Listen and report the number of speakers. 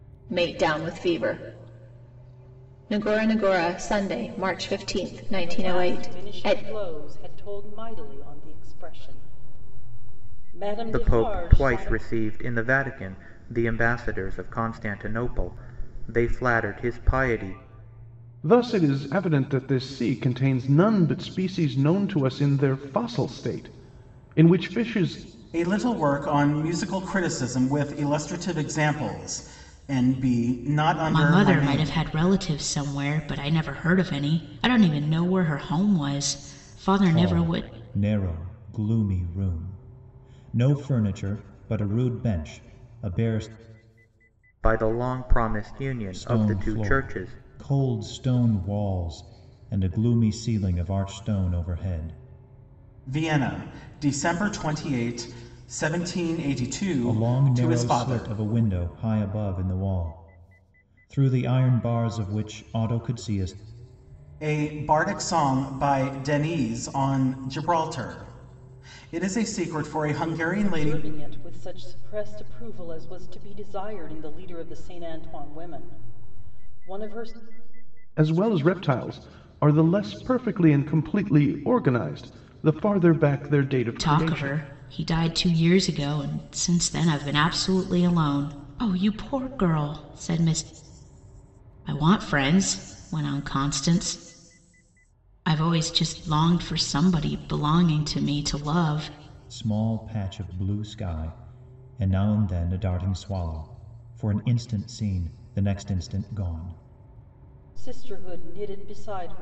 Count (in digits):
7